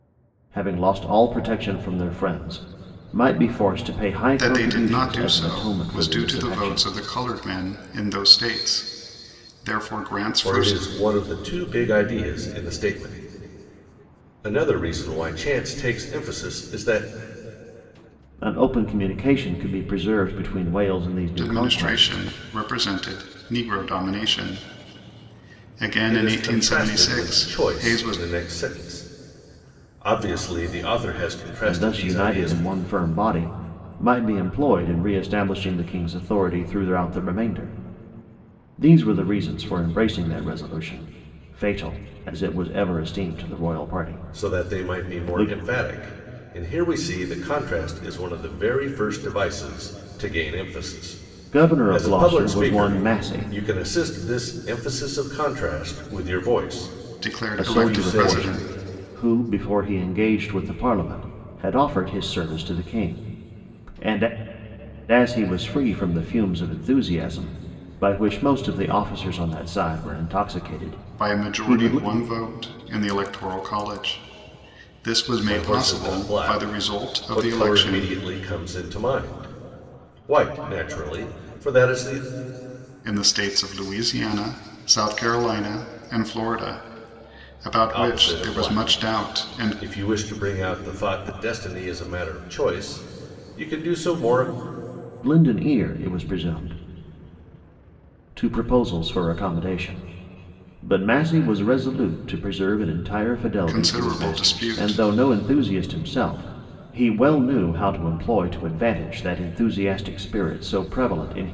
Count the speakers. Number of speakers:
3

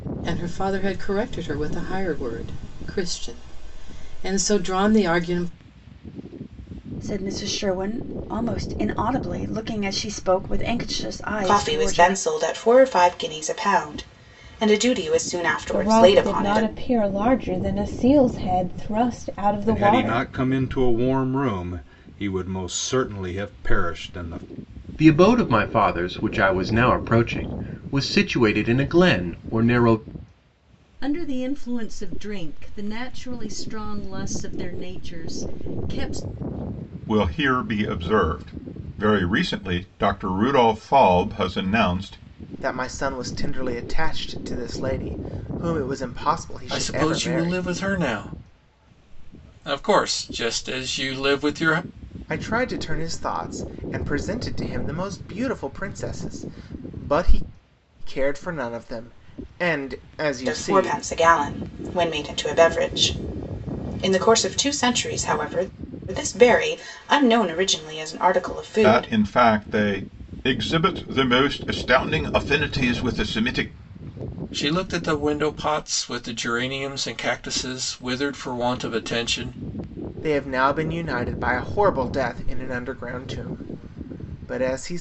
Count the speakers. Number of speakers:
10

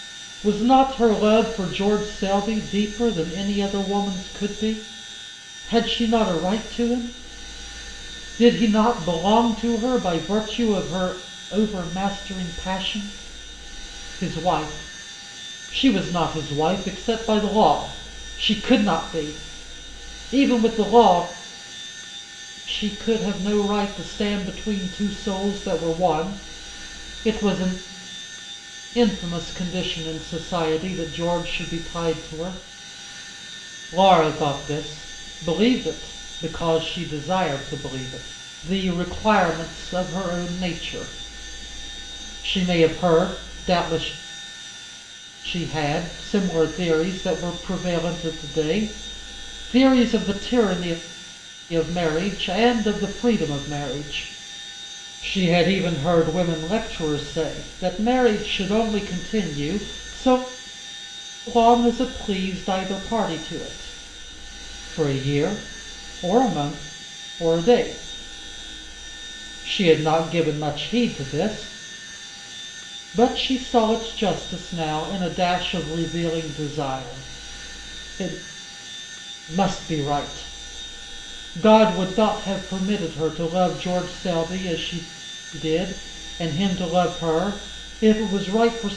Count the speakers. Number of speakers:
1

